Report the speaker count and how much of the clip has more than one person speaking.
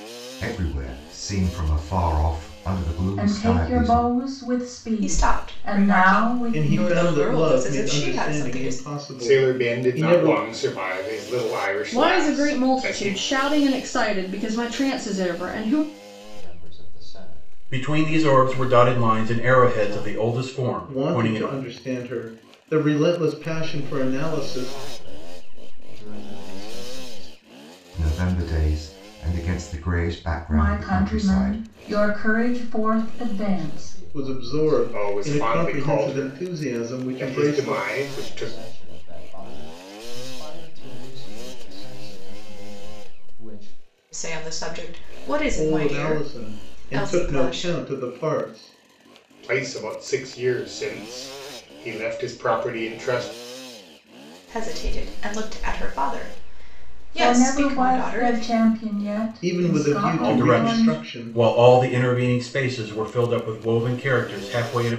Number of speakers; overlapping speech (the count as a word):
eight, about 39%